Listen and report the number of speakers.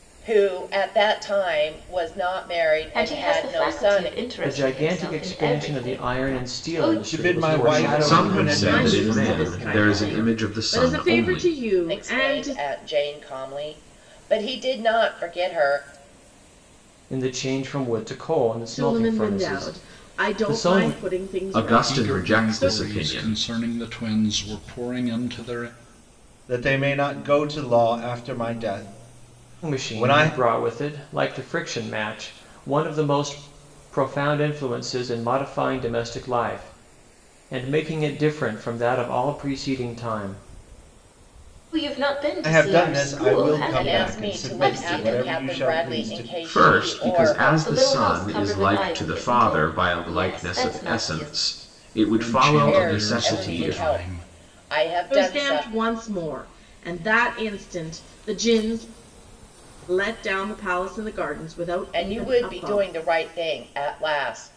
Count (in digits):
7